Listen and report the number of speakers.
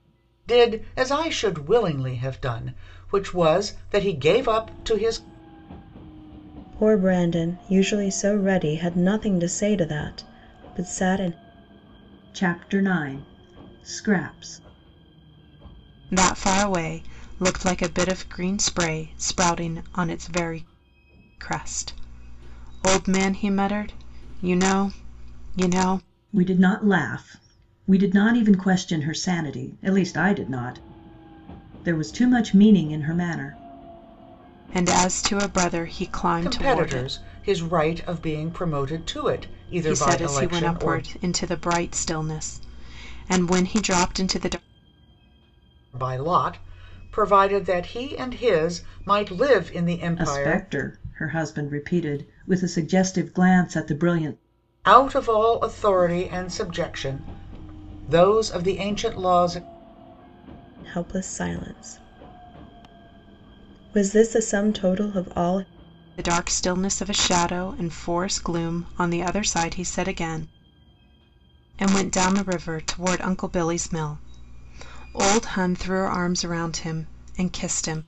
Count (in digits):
4